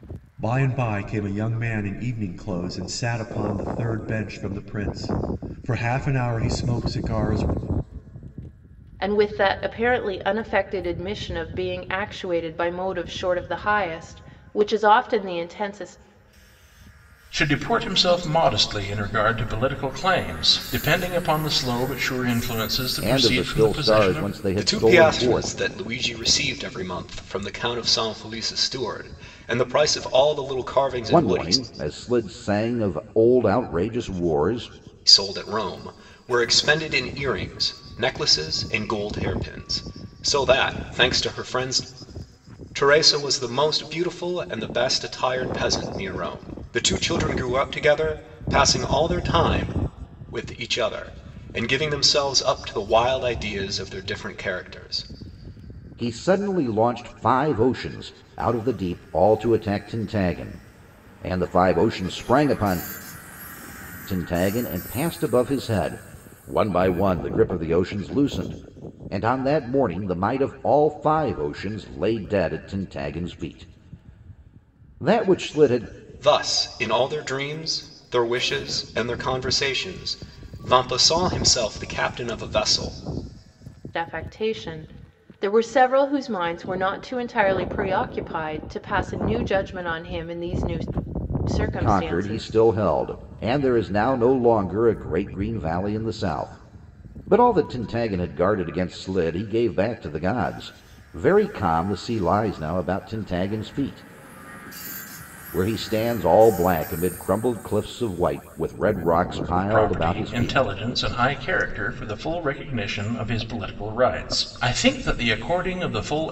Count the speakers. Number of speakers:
five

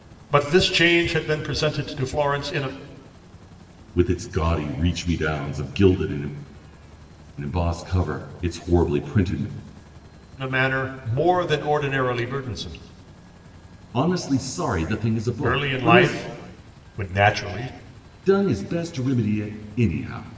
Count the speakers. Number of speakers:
two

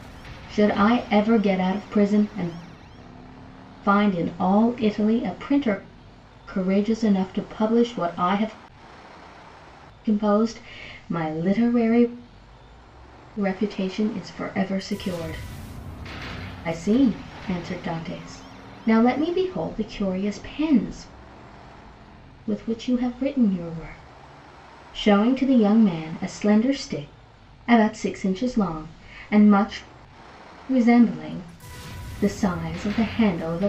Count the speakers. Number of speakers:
one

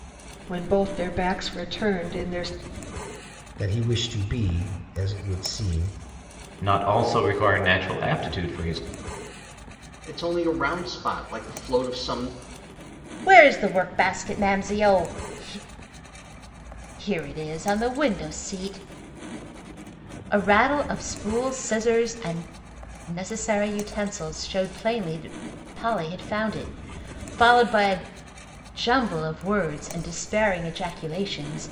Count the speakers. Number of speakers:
five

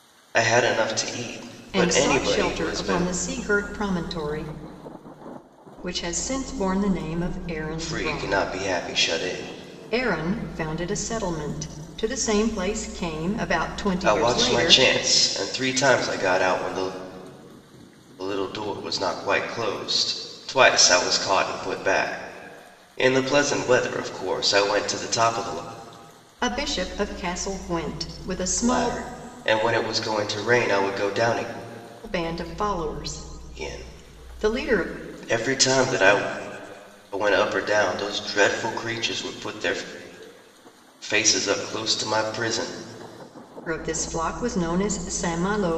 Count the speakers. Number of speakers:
two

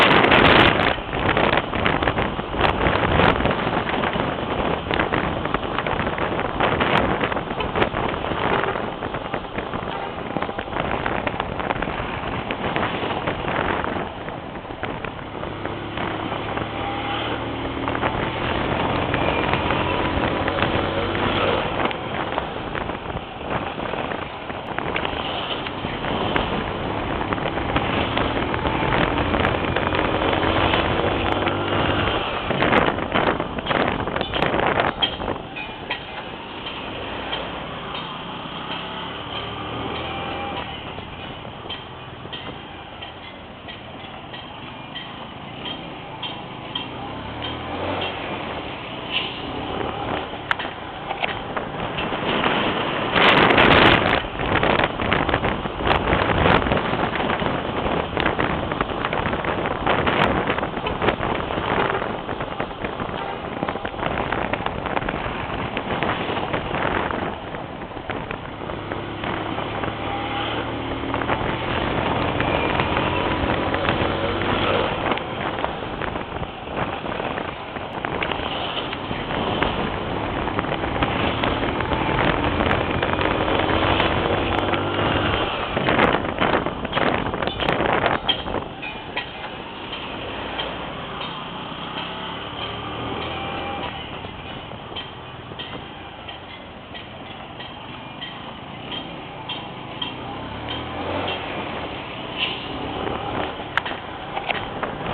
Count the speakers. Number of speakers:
zero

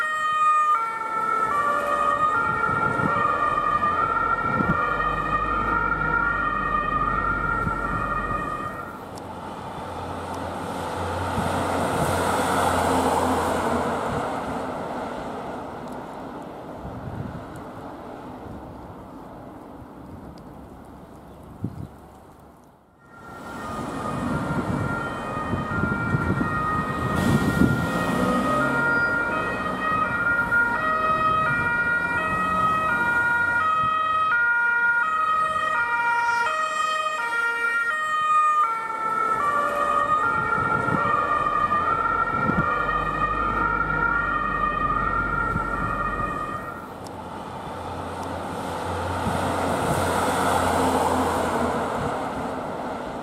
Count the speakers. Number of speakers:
zero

